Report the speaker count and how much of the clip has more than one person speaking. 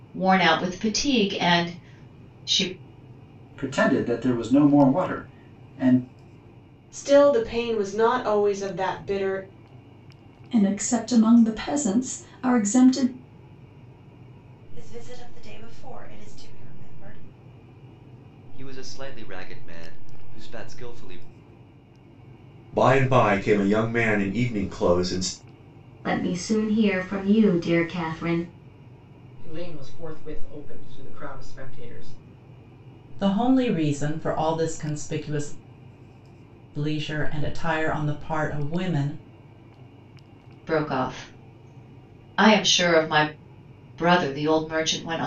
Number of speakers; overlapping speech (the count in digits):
10, no overlap